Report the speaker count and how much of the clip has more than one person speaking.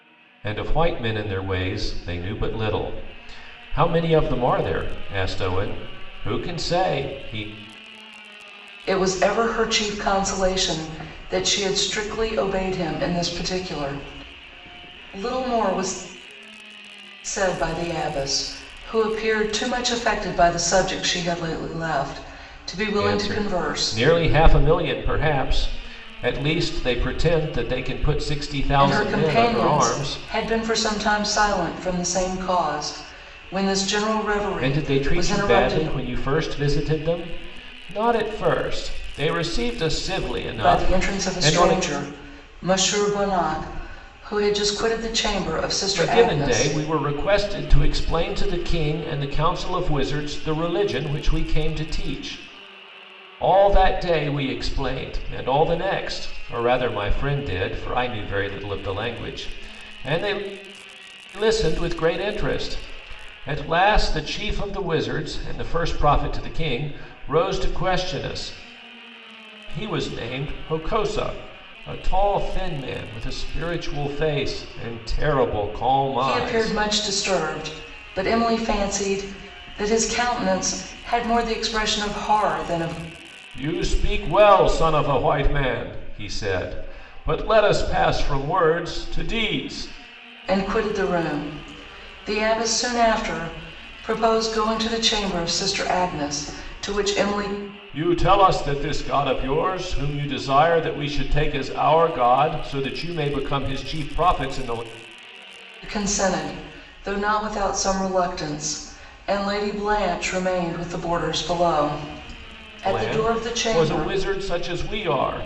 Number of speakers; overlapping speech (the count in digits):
2, about 7%